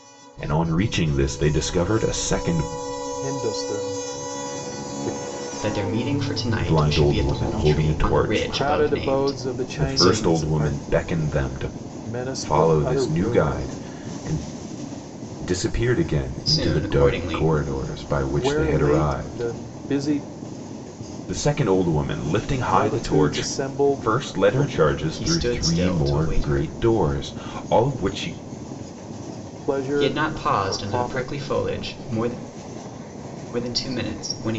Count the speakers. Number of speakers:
3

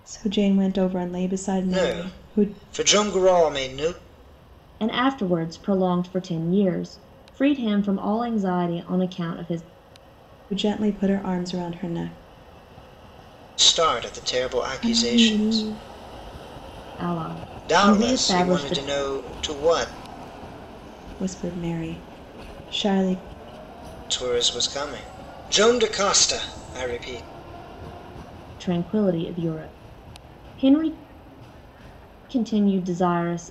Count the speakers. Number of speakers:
3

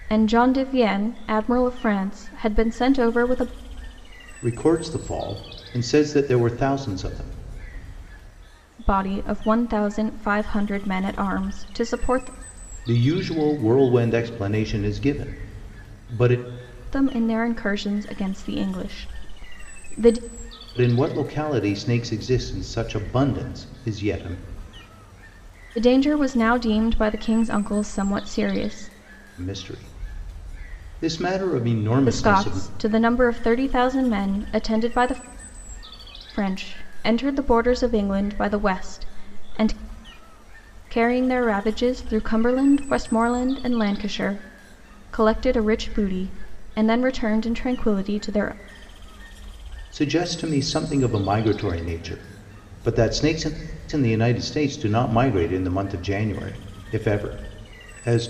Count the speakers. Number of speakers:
2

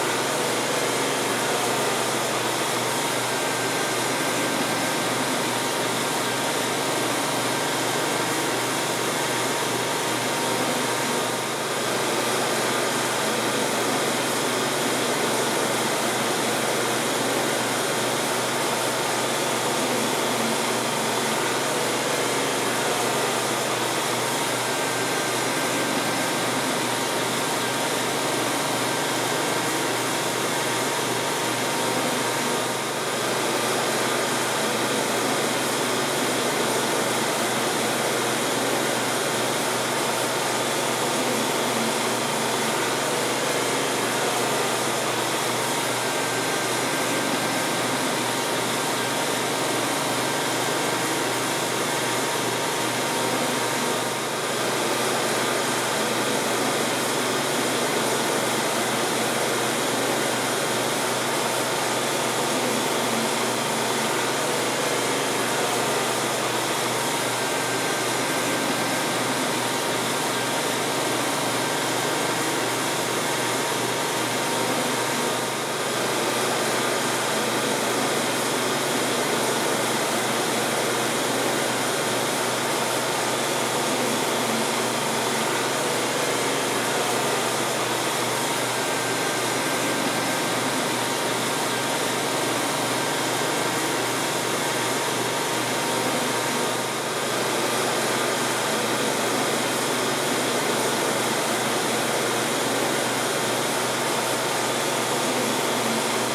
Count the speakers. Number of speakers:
0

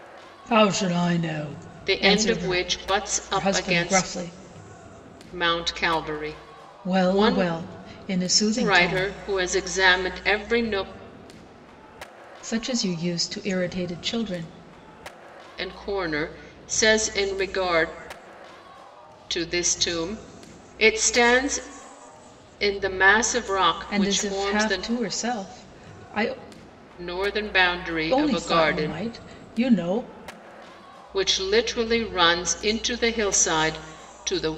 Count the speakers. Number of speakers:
2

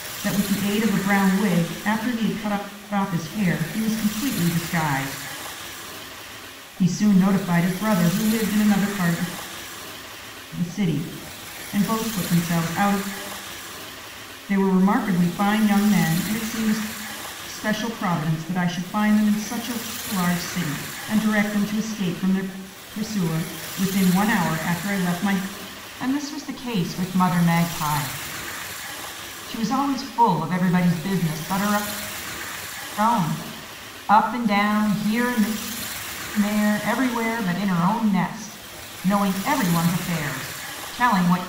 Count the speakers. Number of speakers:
1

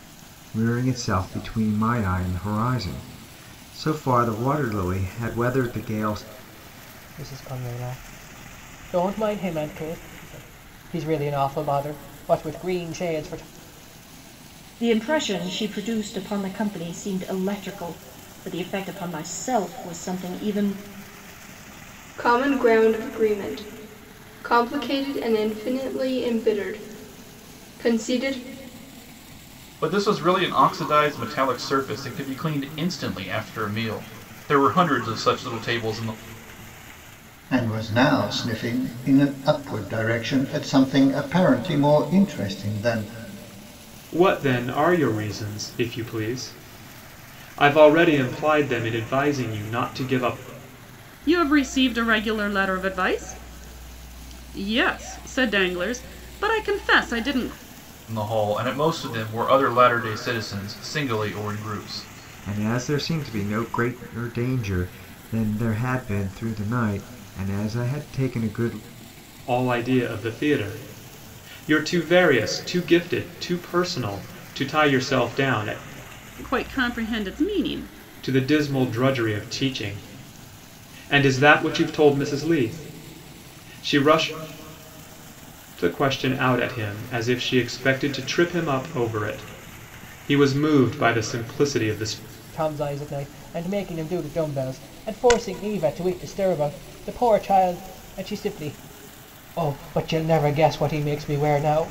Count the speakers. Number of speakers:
8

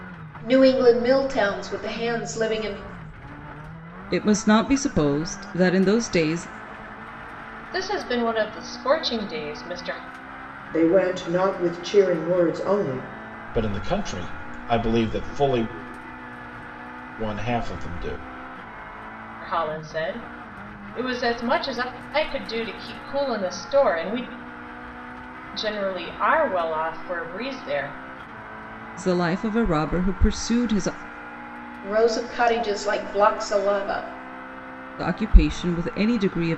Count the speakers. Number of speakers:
5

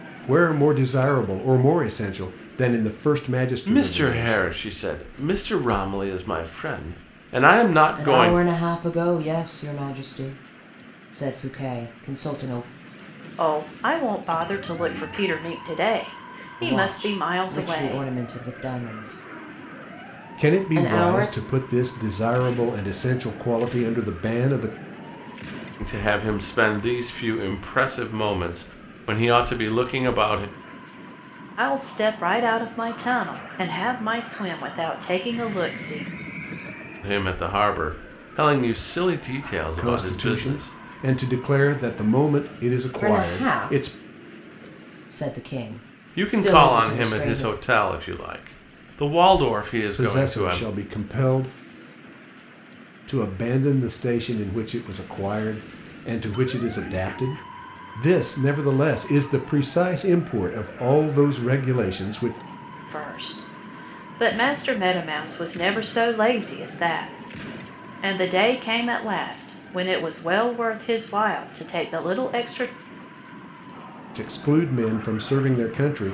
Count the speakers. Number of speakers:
4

